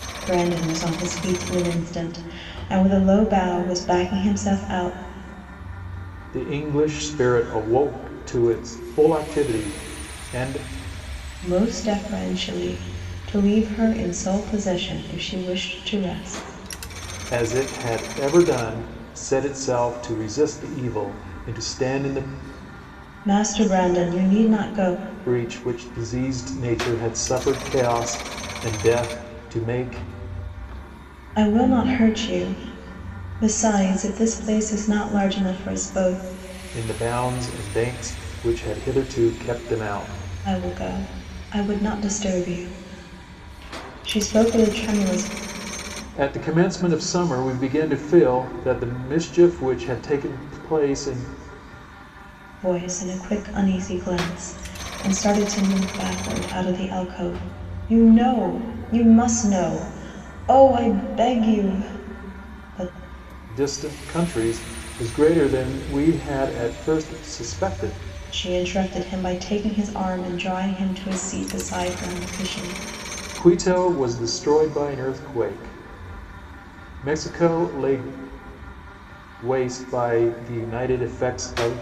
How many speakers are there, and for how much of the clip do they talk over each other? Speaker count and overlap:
two, no overlap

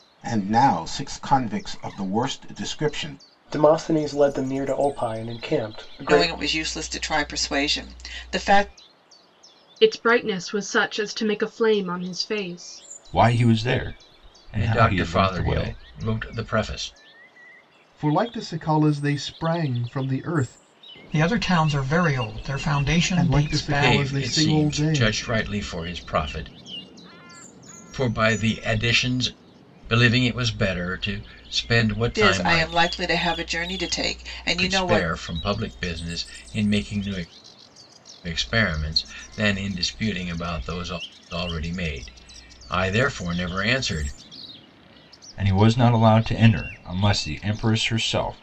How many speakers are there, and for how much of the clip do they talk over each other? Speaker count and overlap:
eight, about 10%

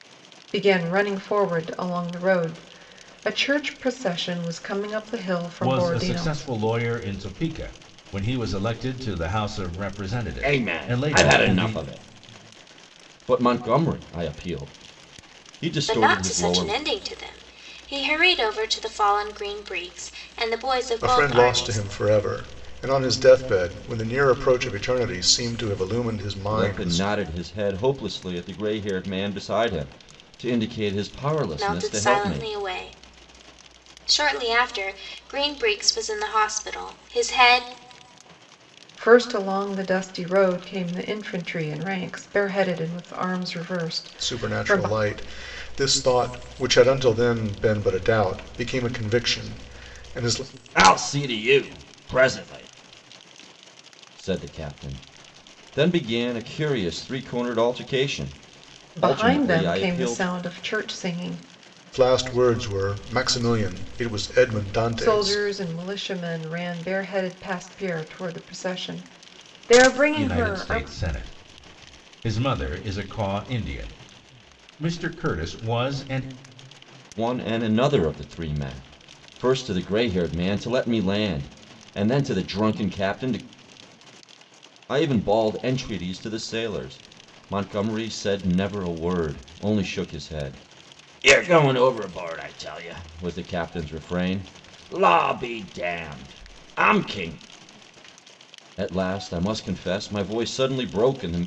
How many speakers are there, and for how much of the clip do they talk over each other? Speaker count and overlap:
five, about 9%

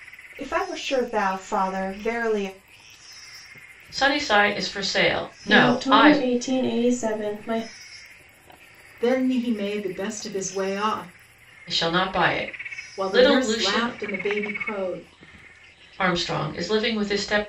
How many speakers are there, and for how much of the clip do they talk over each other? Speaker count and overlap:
four, about 10%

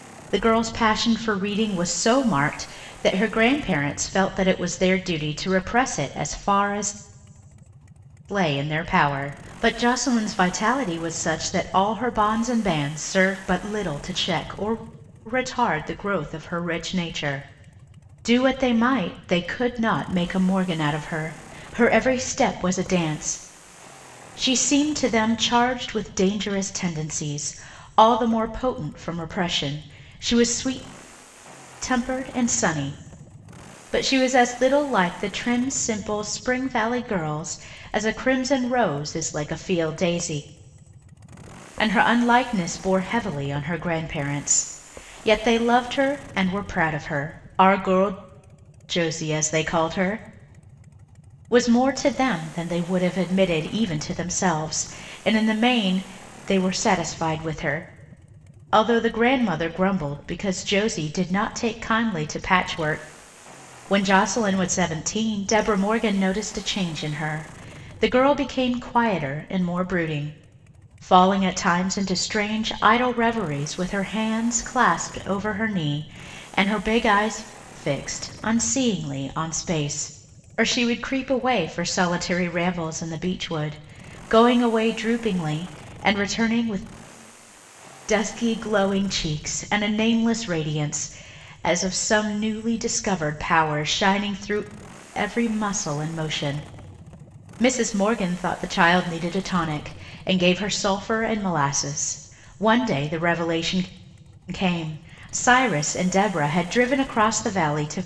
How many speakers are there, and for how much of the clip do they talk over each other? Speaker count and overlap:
one, no overlap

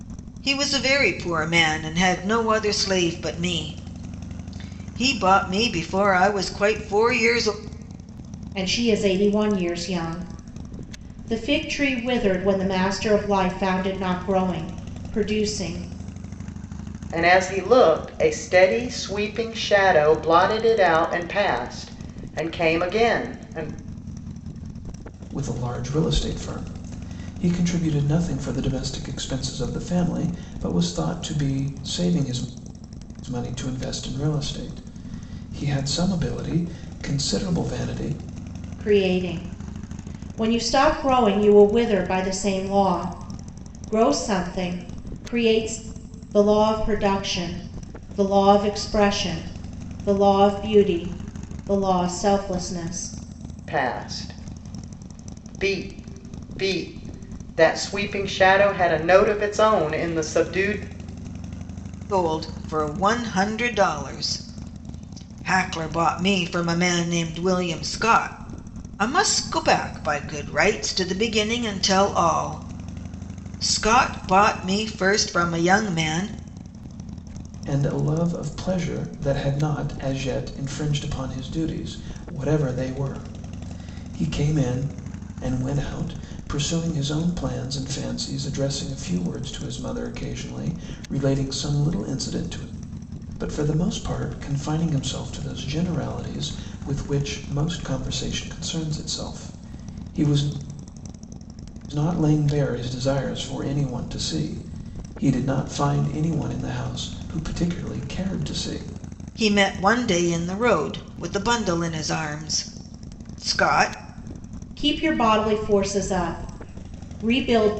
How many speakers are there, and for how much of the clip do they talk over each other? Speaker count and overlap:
four, no overlap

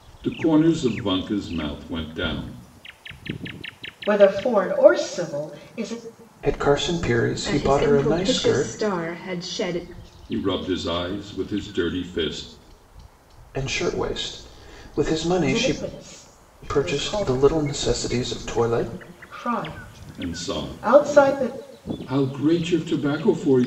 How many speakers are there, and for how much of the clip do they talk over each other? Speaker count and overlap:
four, about 17%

